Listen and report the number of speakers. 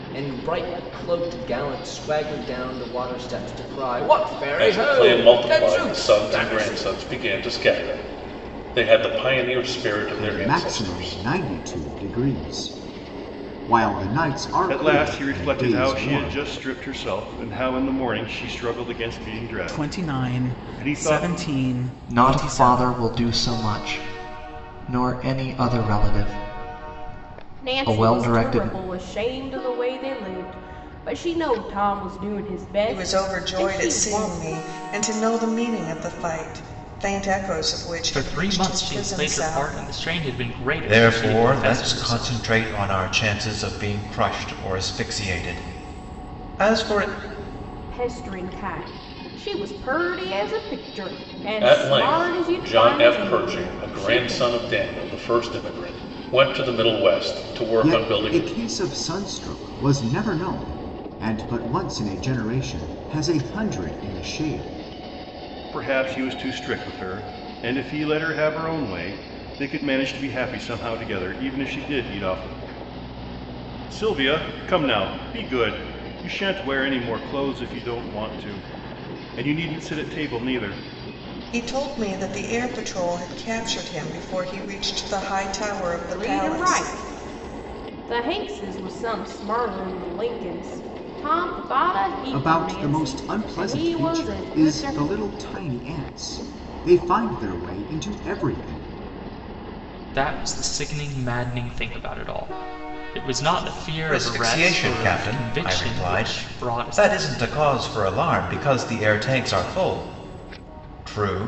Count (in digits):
10